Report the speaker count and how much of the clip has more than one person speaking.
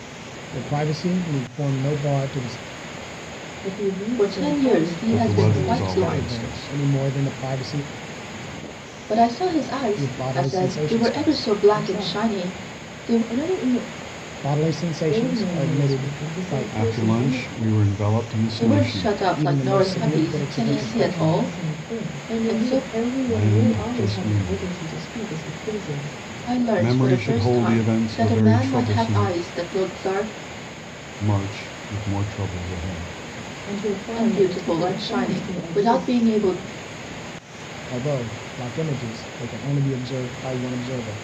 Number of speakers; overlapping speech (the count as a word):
four, about 44%